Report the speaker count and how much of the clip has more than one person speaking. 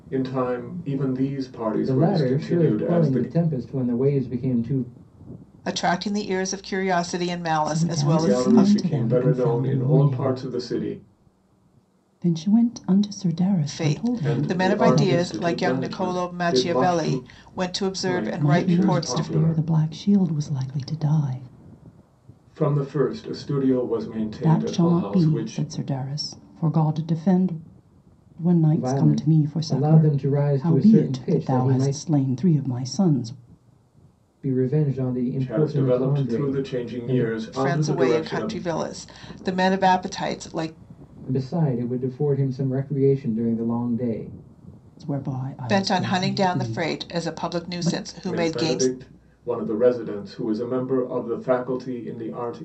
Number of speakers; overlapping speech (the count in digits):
4, about 37%